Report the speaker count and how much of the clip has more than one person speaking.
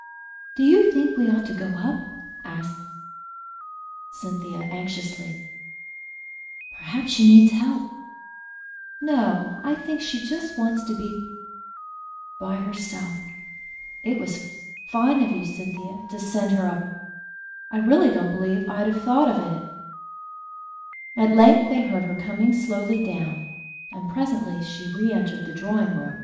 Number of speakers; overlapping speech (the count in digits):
1, no overlap